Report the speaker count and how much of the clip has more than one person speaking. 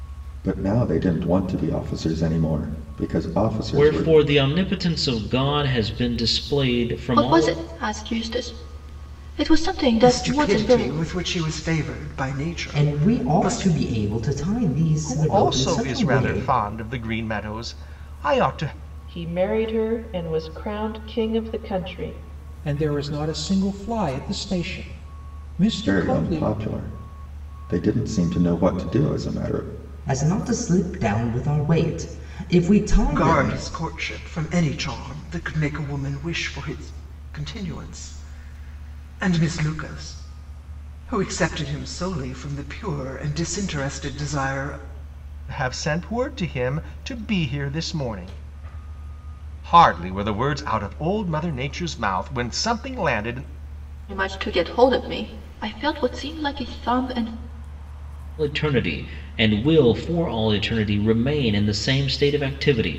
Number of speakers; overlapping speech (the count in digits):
8, about 9%